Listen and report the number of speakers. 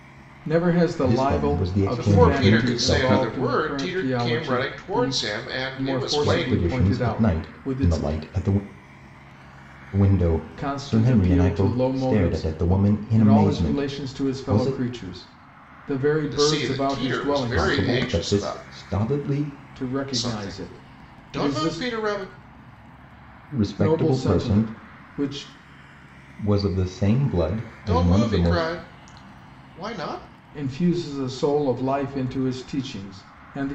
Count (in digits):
3